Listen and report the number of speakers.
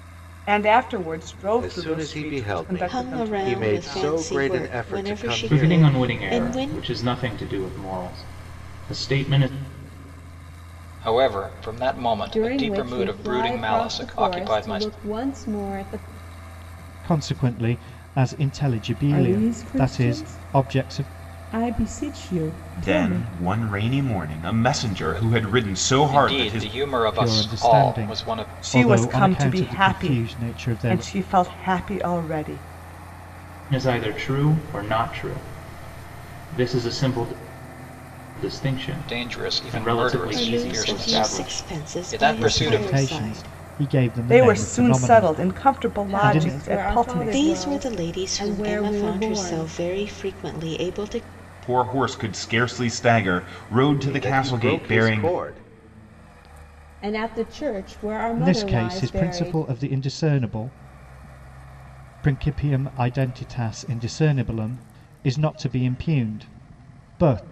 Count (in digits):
9